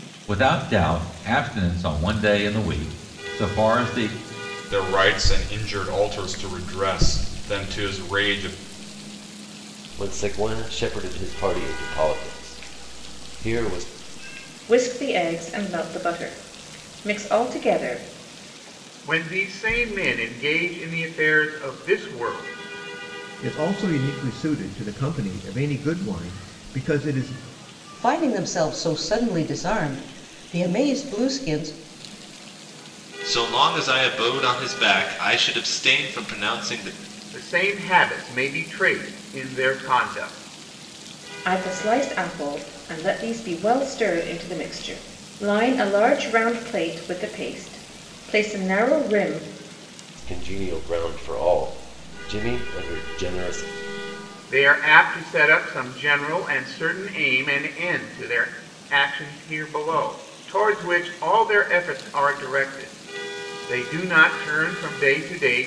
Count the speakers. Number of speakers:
8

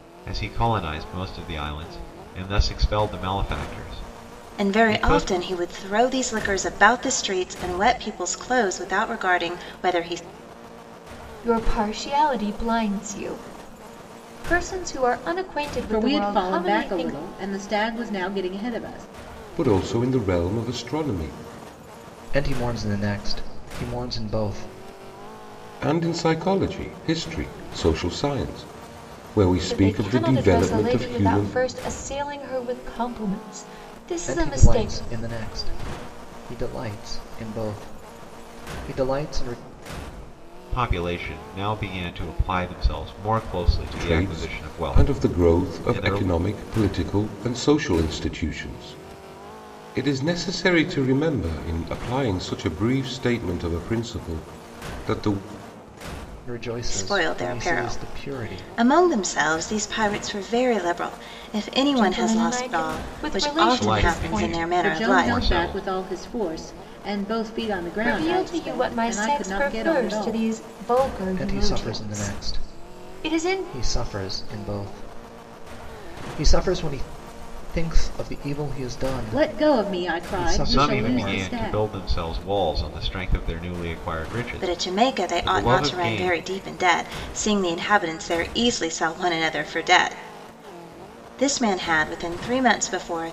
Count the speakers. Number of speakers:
6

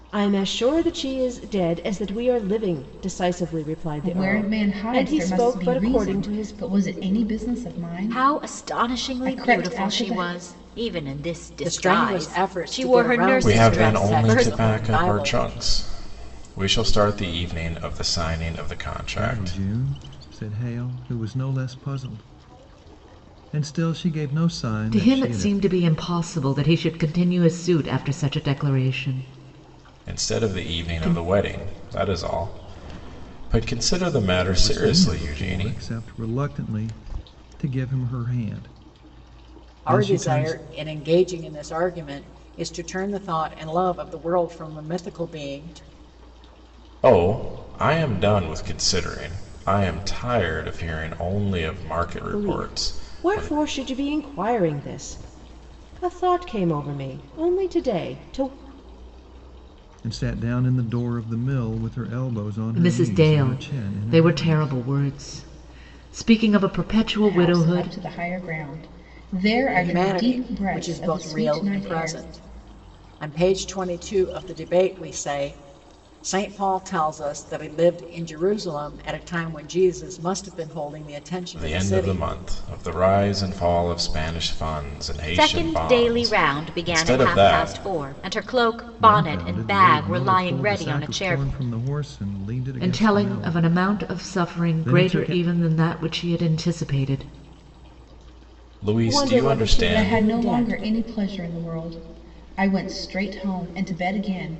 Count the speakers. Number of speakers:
7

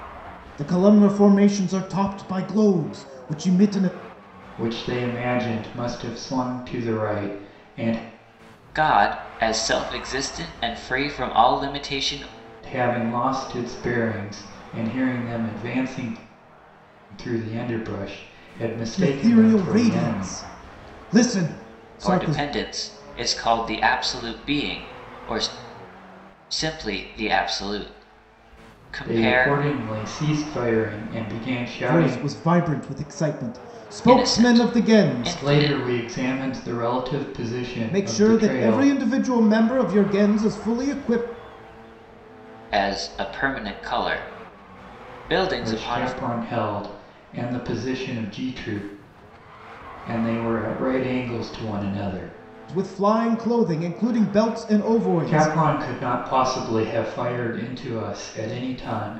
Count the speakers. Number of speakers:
3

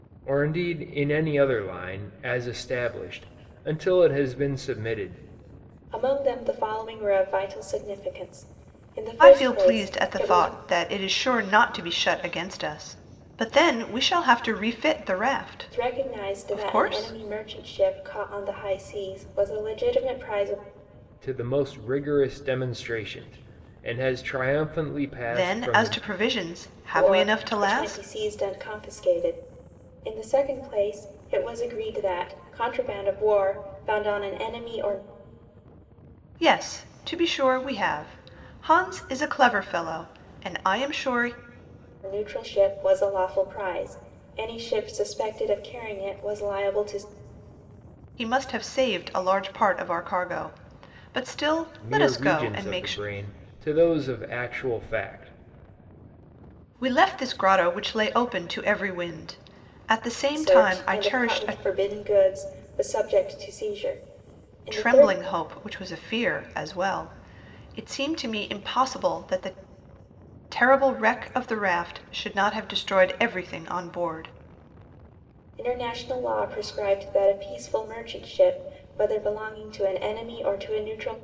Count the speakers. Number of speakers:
3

